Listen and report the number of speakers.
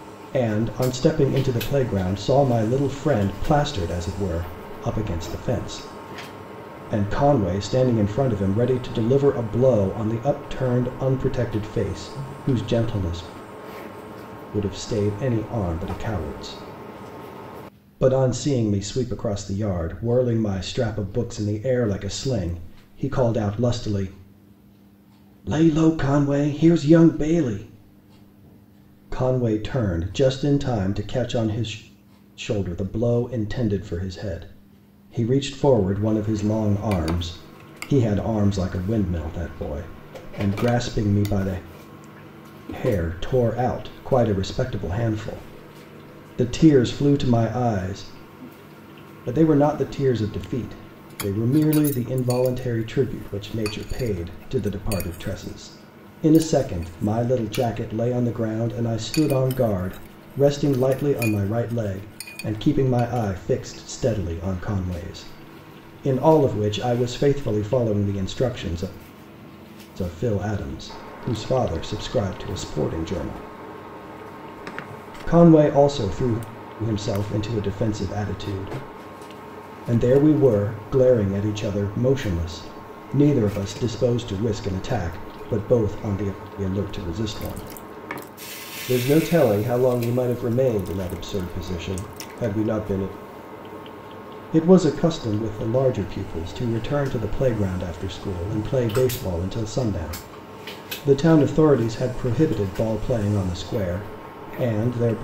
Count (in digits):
1